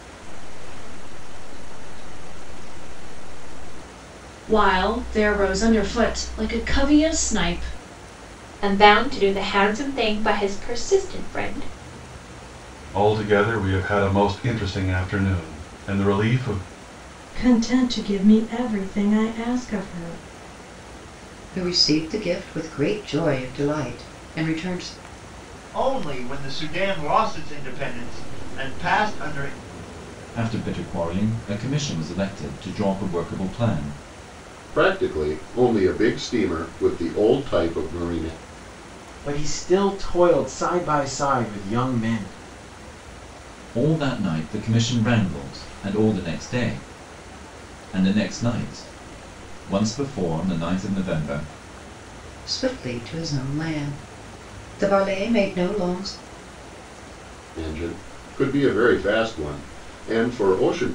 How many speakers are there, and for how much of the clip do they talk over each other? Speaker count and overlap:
10, no overlap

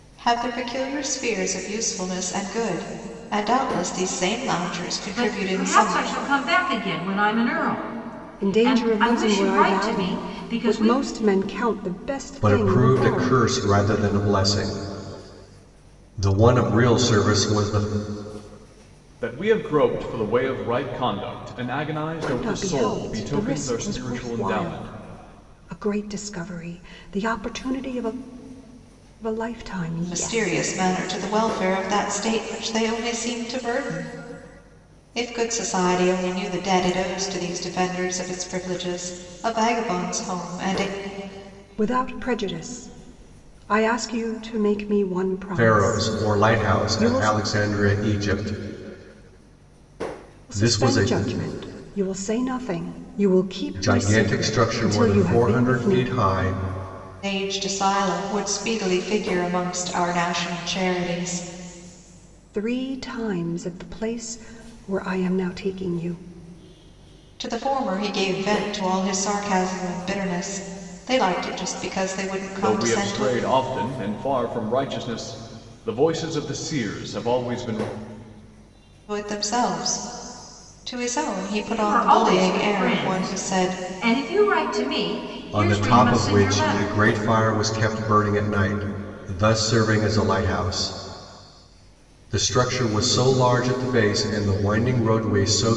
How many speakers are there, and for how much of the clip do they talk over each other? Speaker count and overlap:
5, about 18%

